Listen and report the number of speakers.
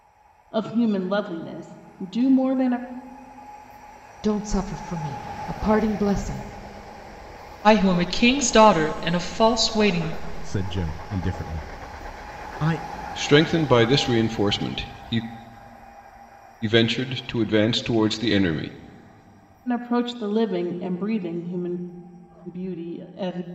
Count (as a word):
five